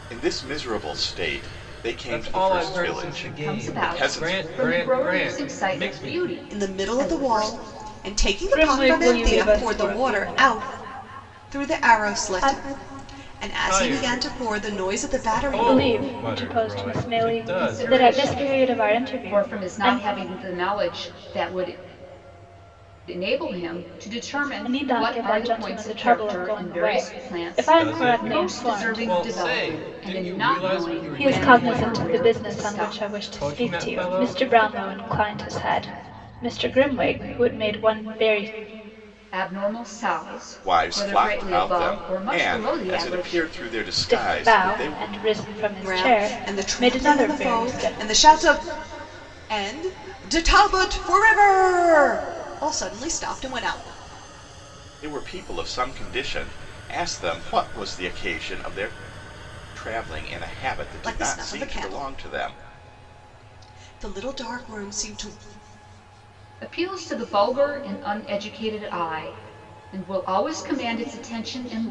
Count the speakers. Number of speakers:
5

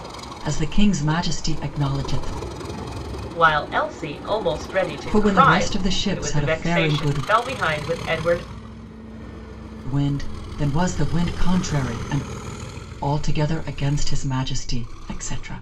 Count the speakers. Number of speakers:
2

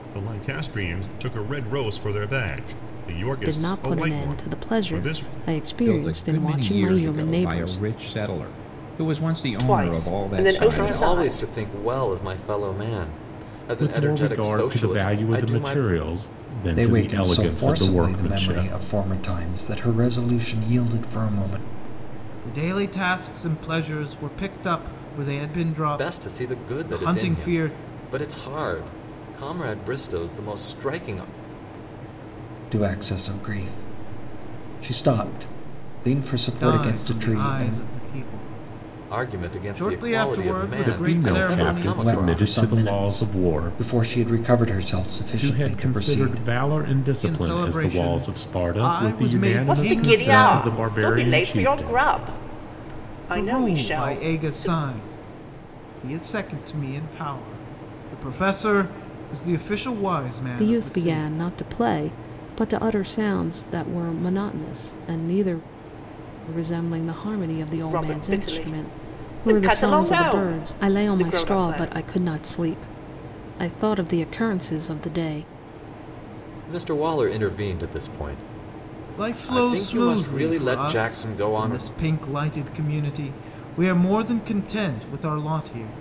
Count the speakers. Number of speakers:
8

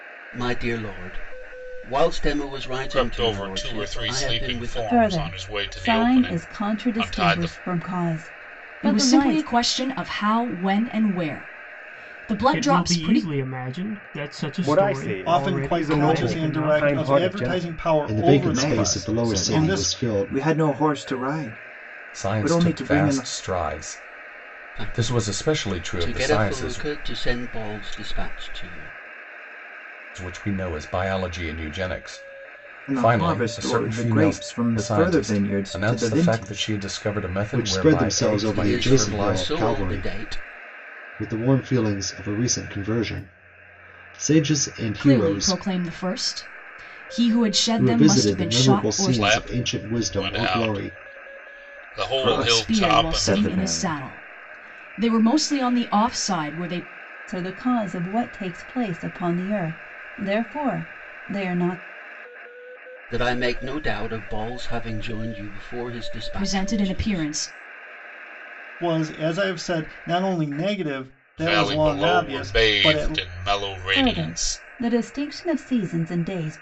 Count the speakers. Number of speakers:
10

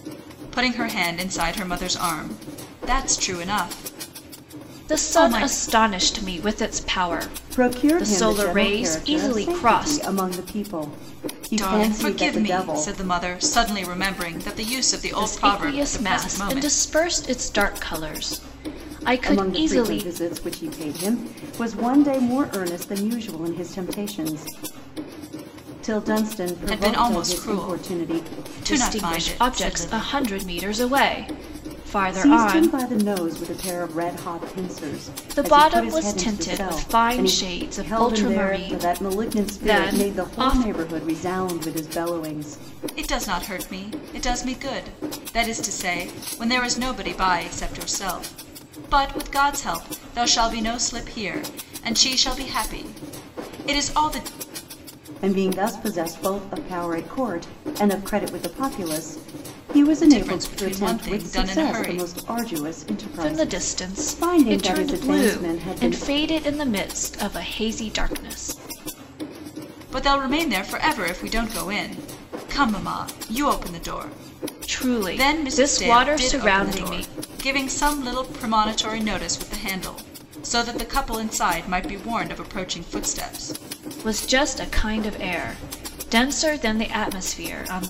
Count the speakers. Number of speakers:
3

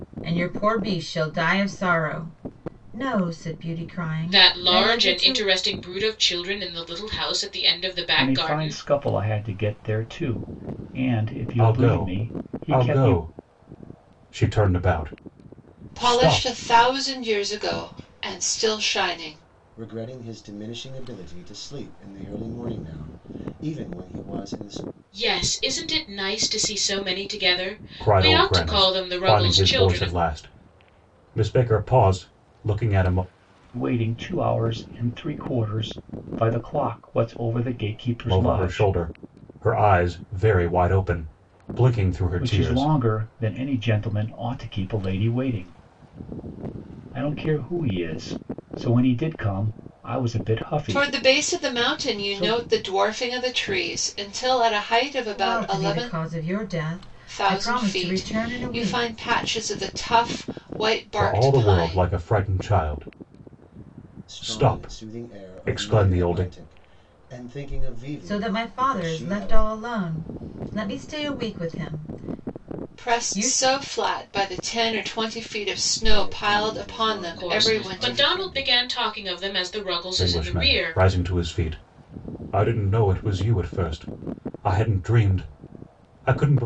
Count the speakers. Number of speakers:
6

